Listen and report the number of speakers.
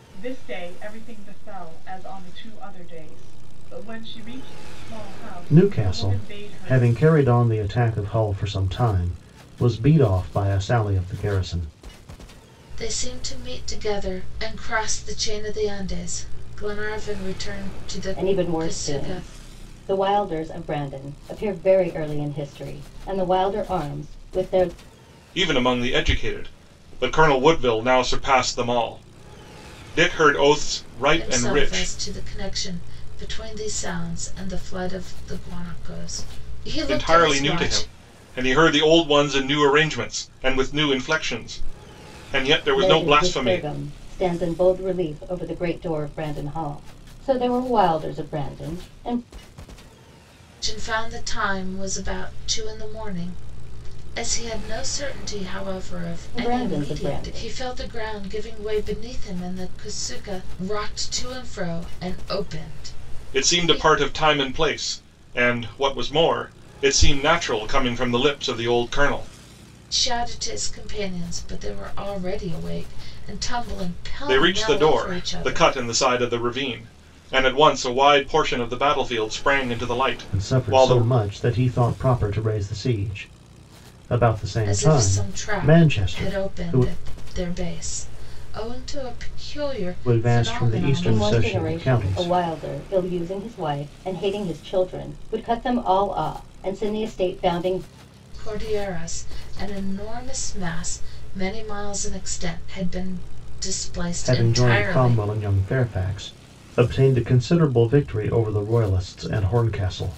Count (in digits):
5